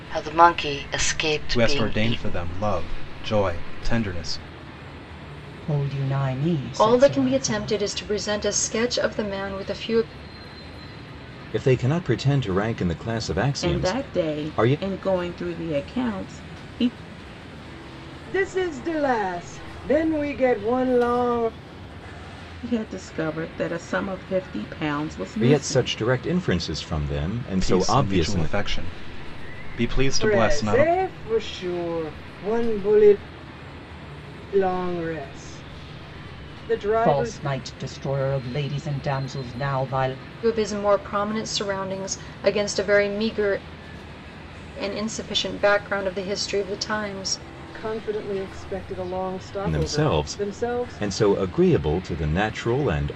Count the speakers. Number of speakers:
7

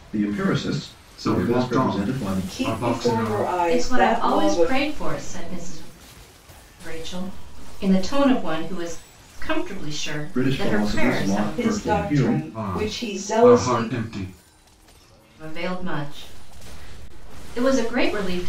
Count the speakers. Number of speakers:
4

